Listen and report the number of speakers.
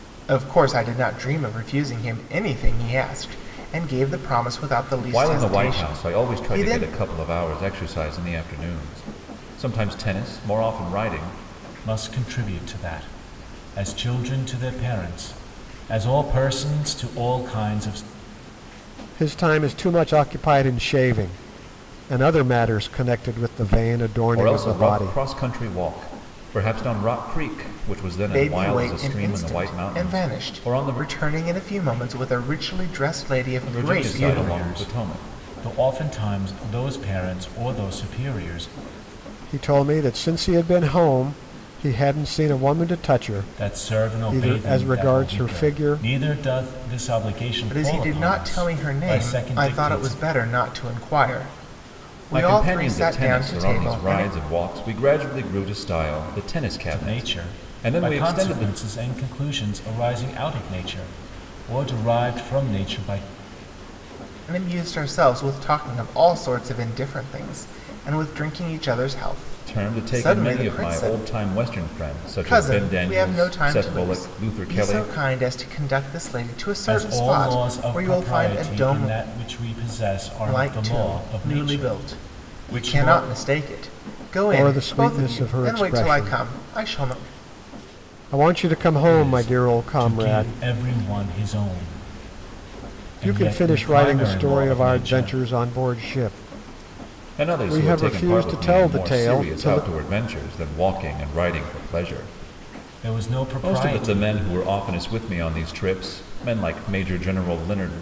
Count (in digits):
4